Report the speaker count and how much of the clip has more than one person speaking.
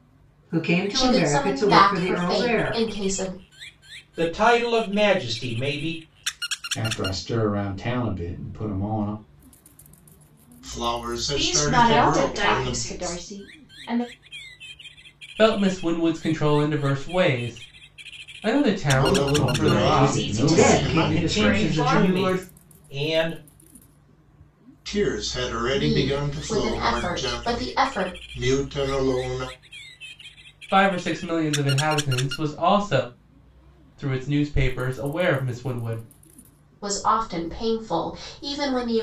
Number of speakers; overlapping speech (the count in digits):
8, about 25%